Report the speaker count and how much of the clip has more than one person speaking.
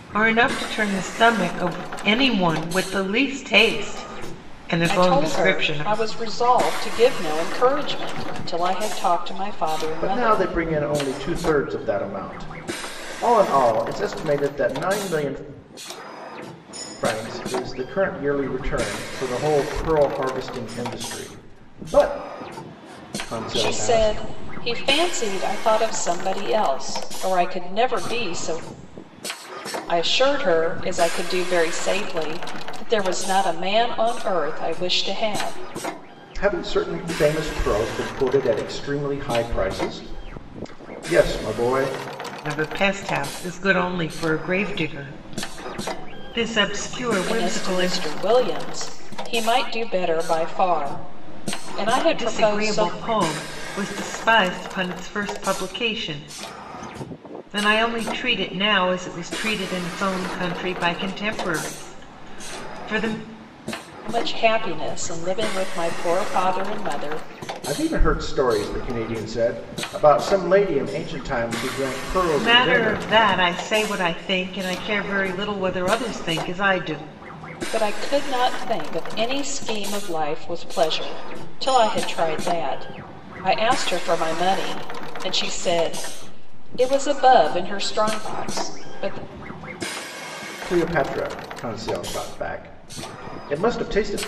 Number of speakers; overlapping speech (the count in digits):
3, about 5%